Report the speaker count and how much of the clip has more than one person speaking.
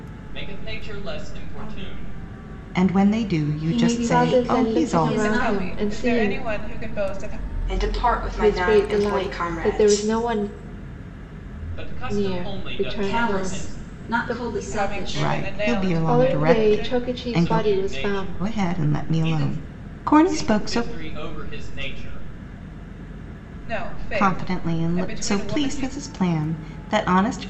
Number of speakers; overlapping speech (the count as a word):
six, about 52%